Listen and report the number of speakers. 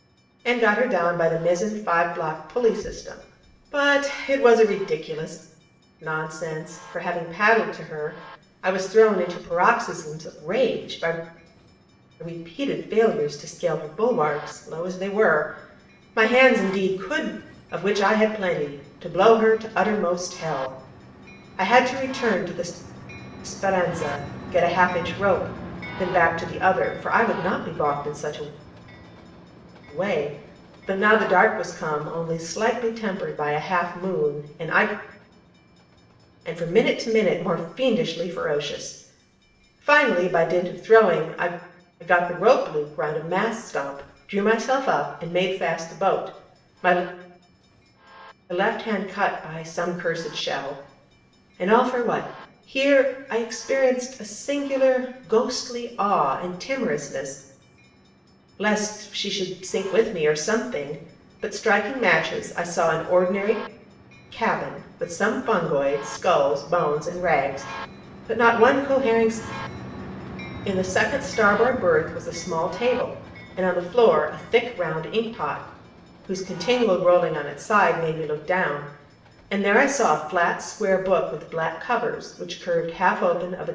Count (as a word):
one